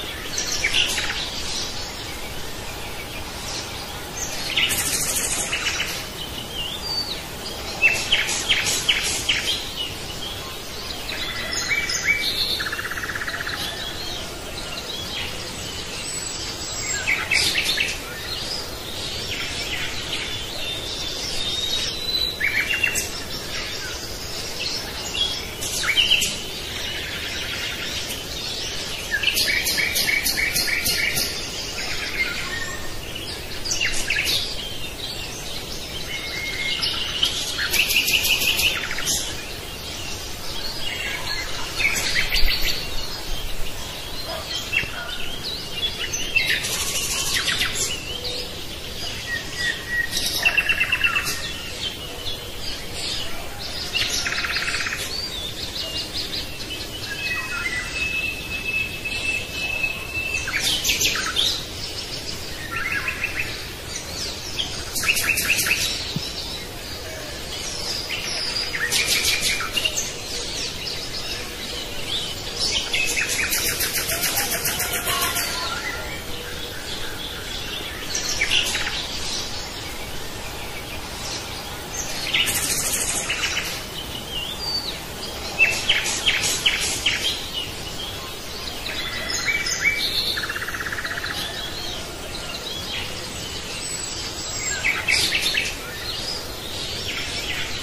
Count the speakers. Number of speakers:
0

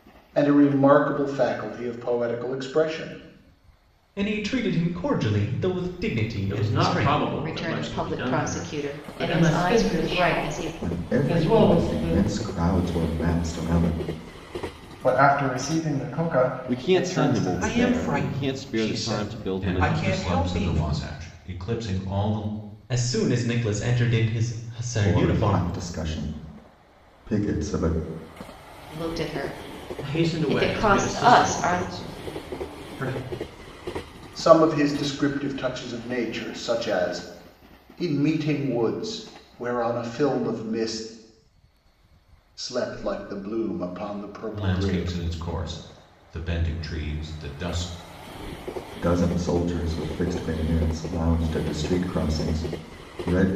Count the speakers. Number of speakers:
10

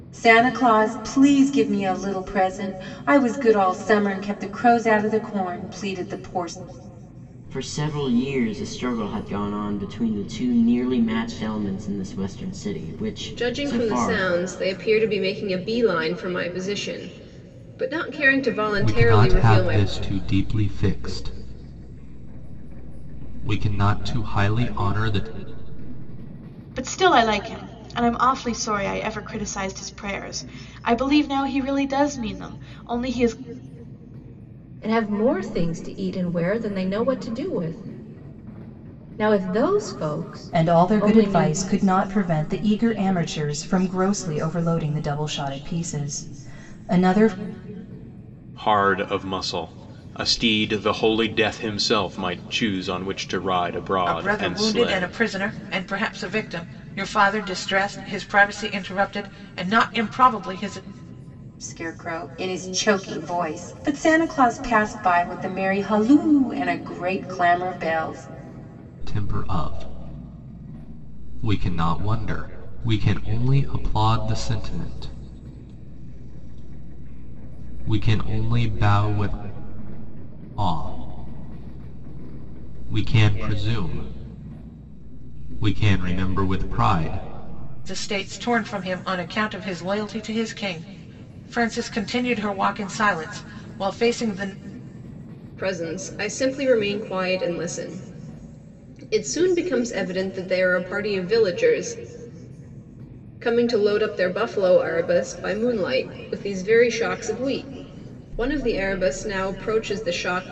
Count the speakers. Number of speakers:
9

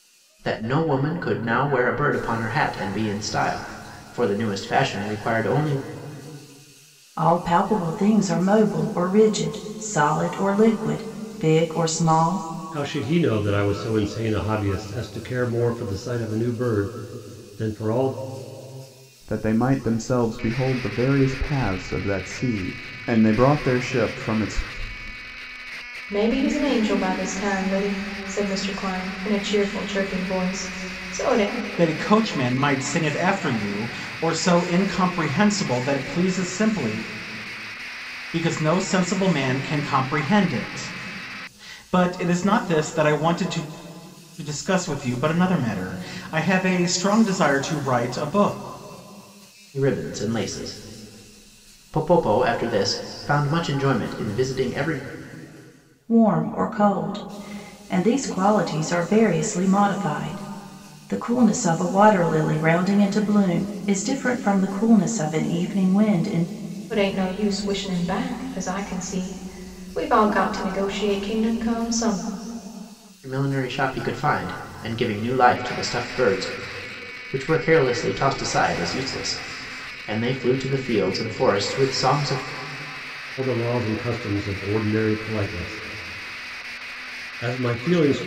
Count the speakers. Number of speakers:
6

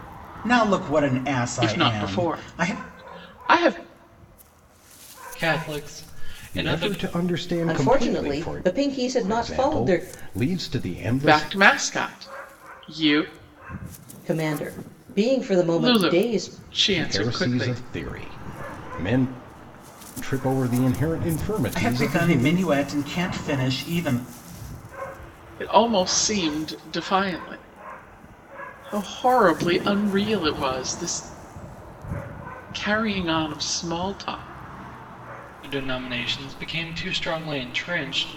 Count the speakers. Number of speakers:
5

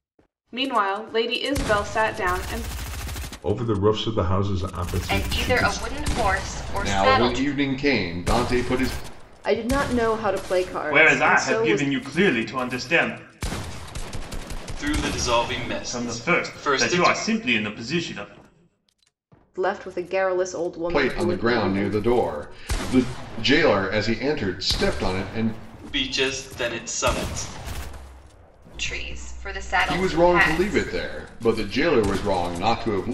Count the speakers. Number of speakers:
7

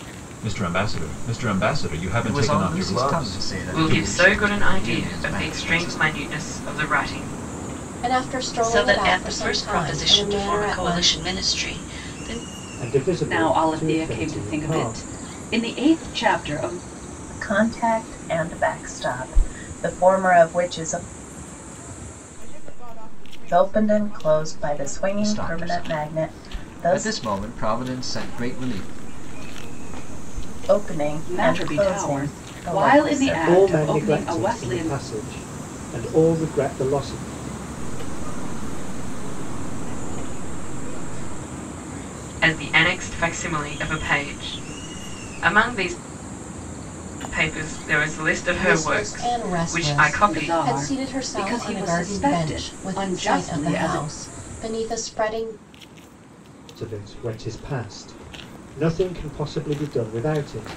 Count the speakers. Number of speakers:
9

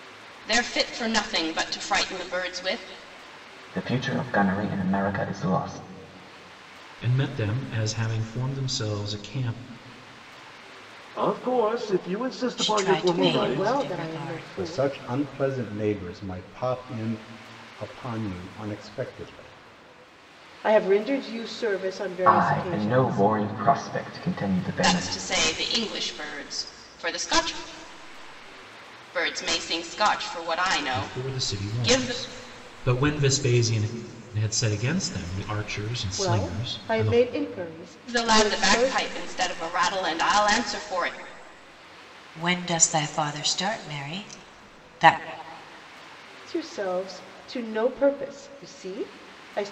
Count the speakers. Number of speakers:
7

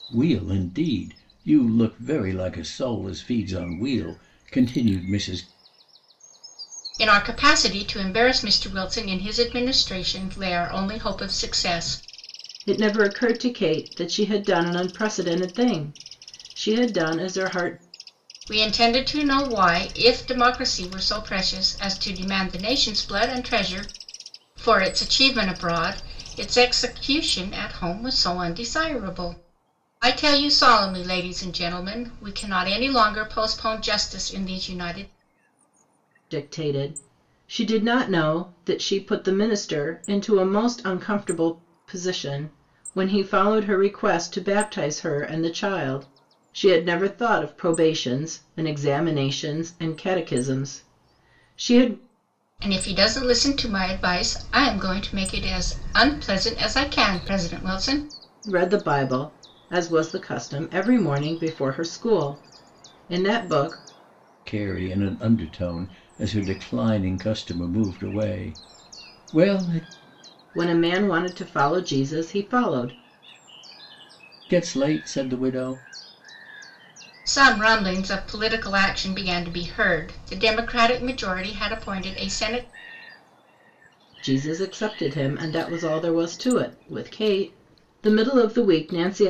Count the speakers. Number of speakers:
3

